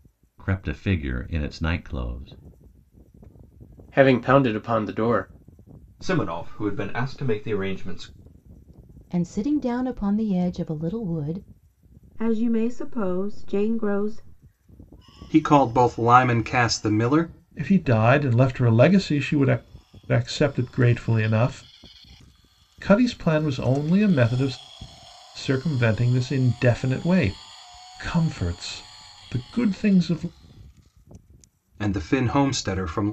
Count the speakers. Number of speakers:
seven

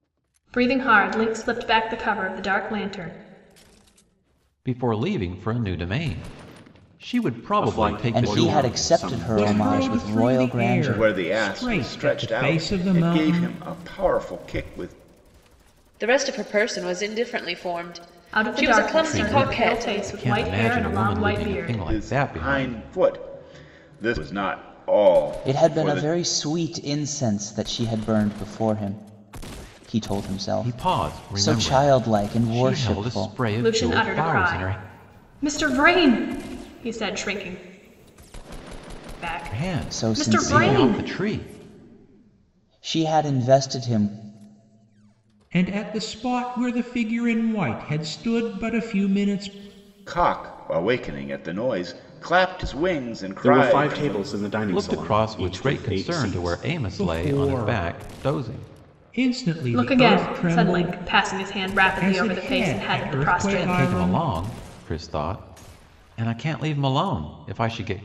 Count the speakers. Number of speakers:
seven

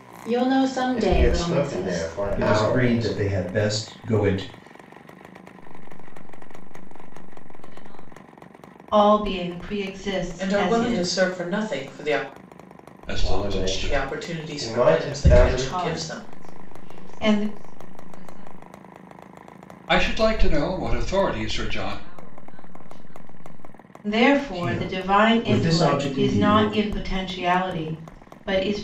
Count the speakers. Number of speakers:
seven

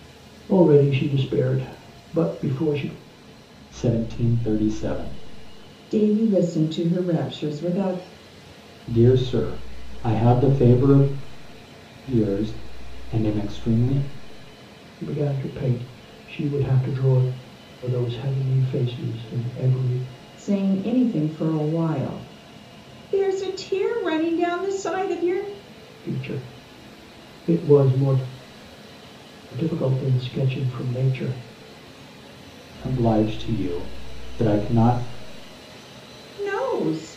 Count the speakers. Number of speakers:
three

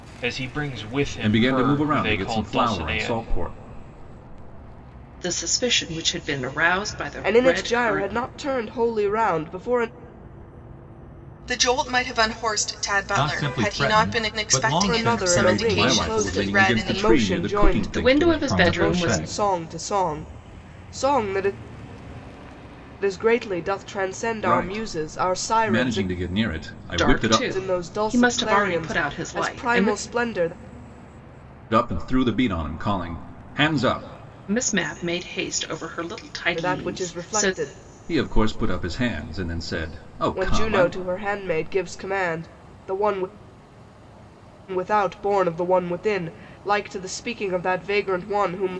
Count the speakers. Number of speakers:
six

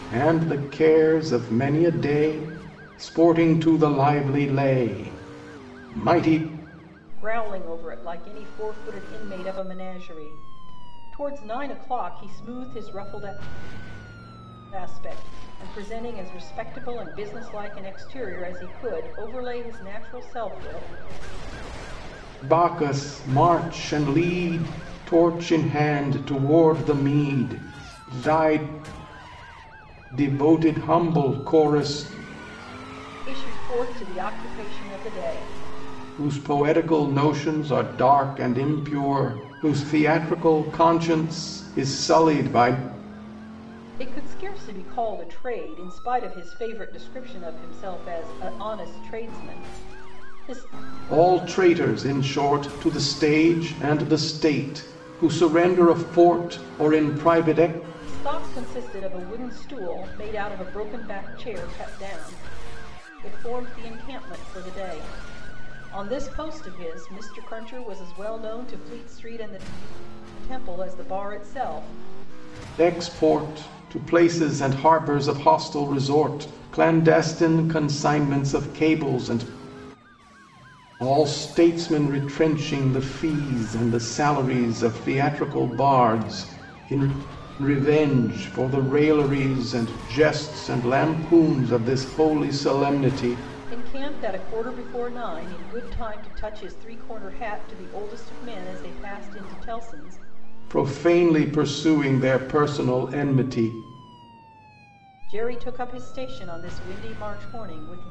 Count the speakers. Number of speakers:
two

